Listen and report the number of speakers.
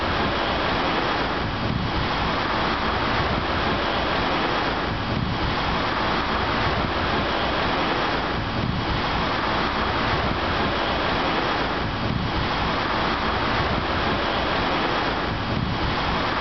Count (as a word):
zero